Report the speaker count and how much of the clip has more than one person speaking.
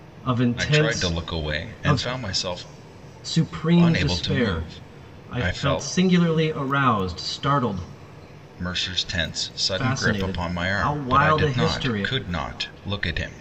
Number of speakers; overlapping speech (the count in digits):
2, about 45%